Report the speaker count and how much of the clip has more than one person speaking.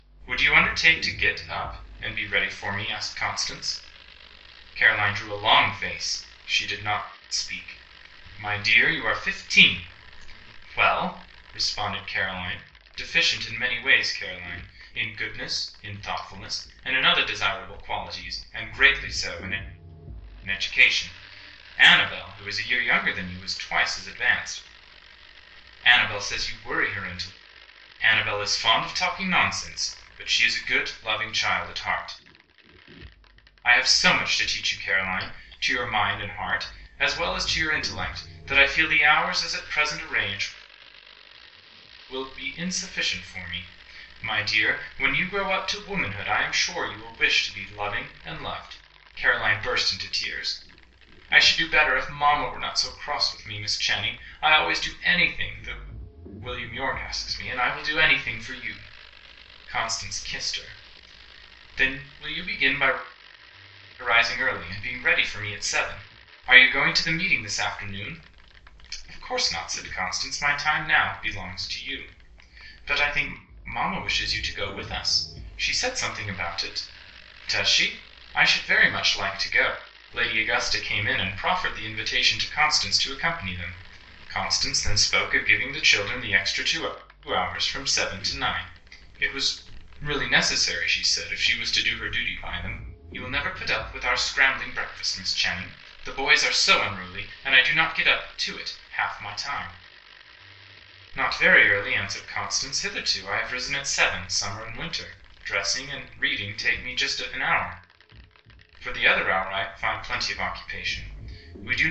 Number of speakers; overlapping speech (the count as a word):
one, no overlap